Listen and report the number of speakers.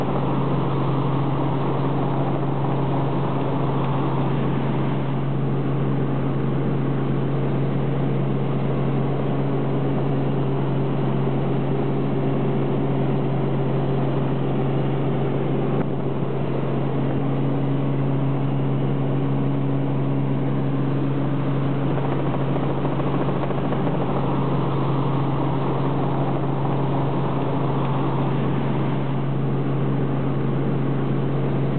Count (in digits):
0